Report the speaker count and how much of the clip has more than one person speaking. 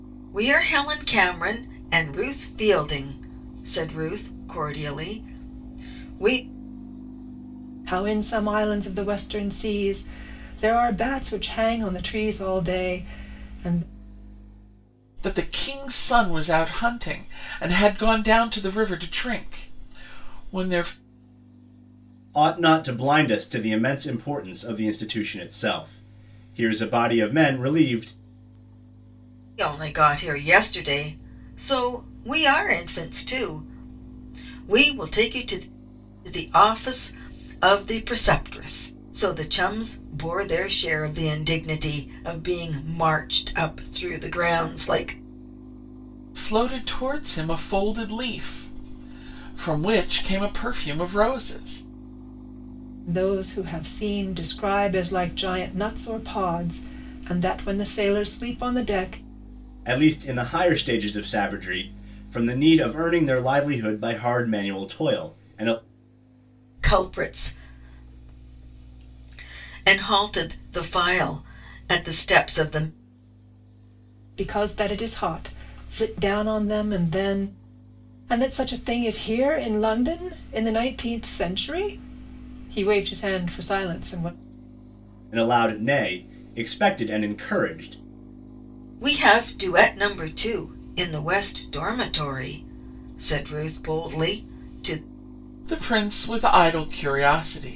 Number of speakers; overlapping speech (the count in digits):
4, no overlap